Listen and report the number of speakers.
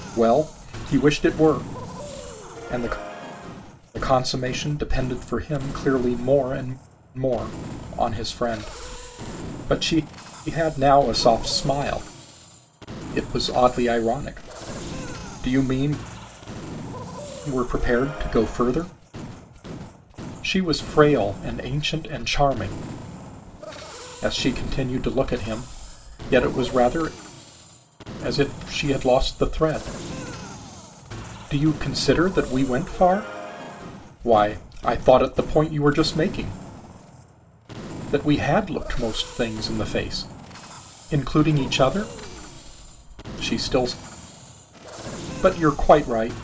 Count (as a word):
one